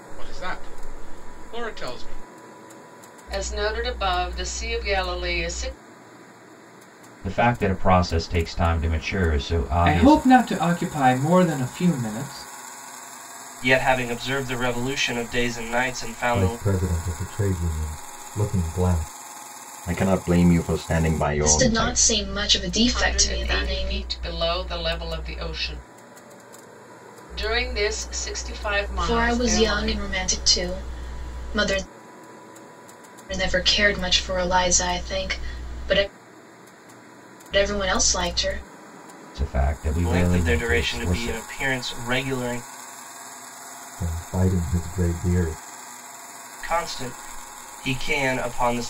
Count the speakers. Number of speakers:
eight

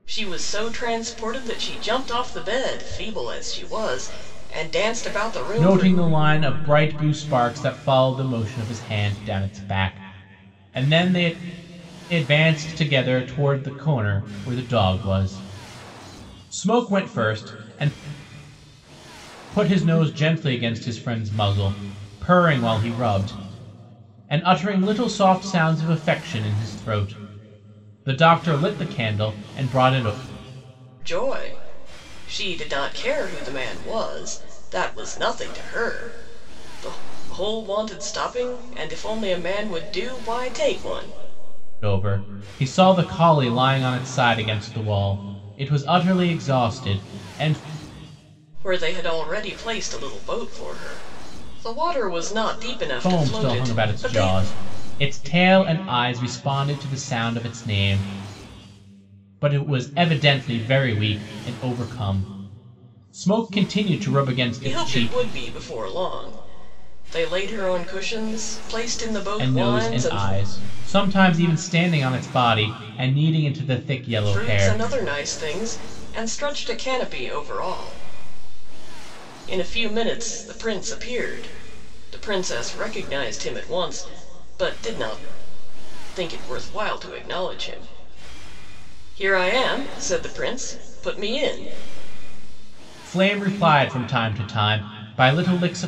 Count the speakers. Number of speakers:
two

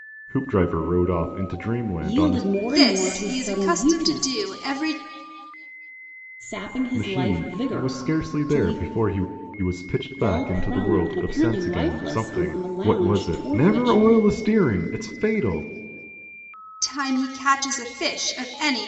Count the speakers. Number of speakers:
three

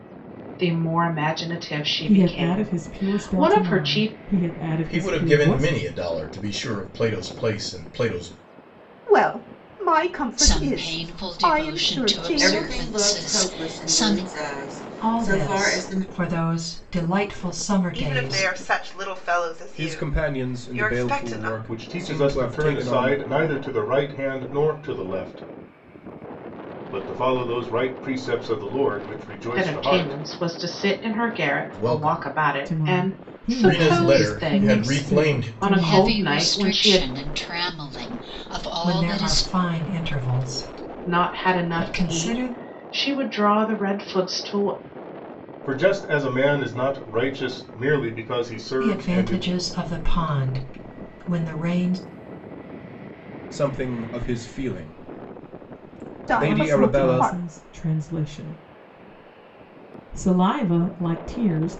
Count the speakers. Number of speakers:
ten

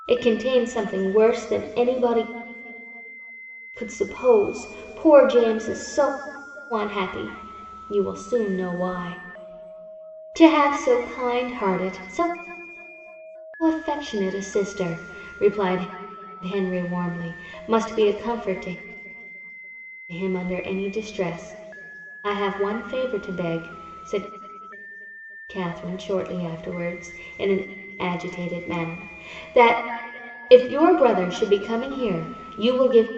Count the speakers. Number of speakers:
one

